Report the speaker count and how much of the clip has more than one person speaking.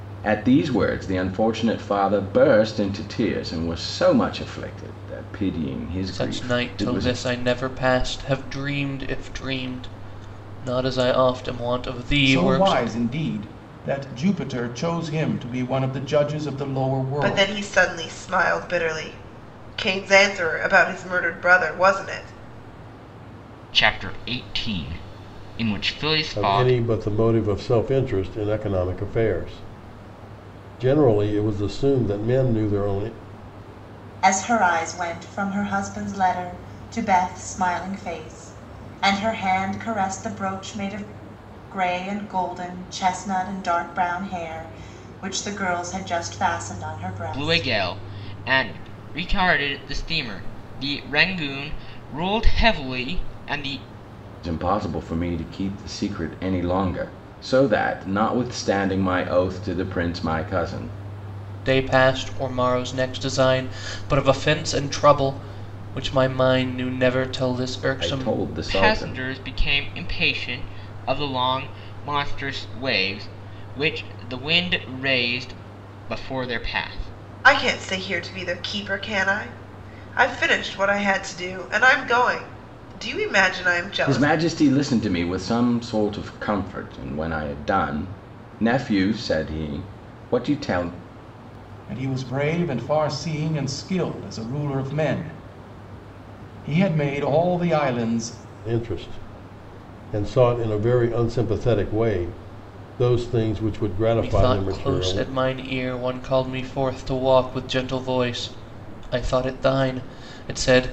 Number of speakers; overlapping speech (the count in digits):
7, about 5%